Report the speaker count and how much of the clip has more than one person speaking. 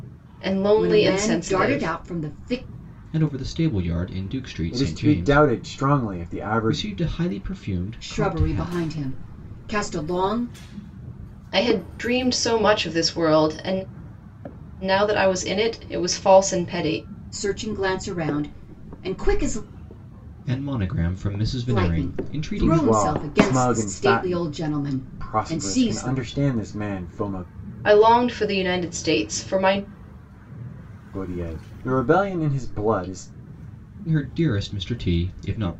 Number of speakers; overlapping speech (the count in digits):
4, about 20%